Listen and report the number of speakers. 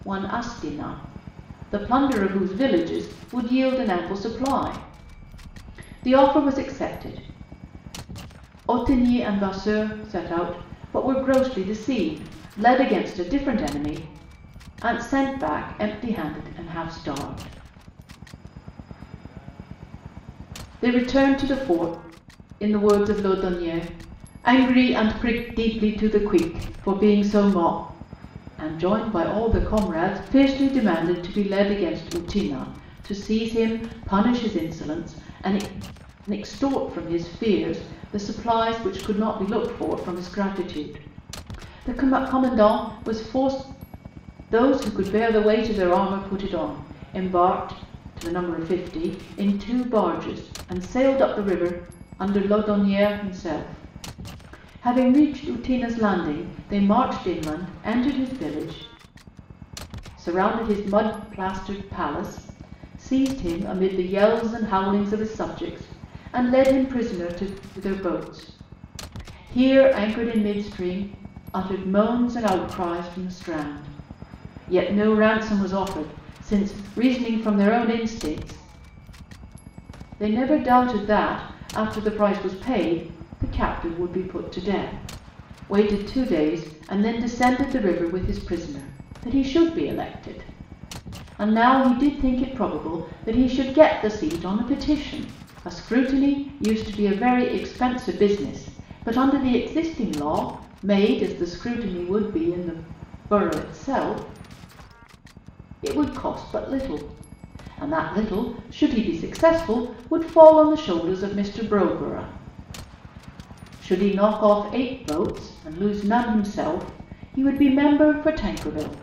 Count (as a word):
one